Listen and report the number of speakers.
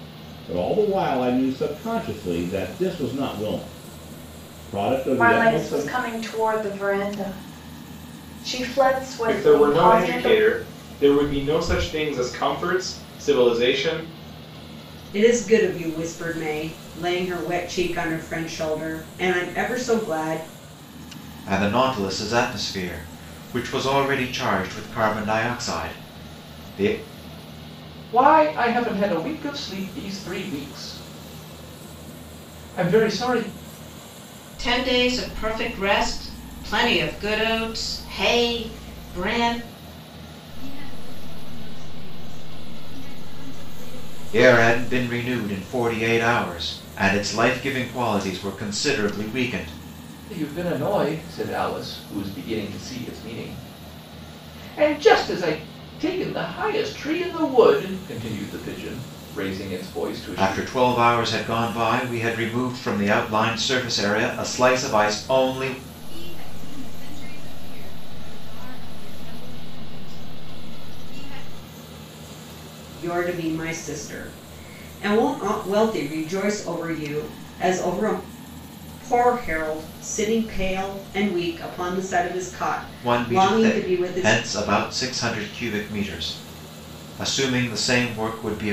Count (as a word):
eight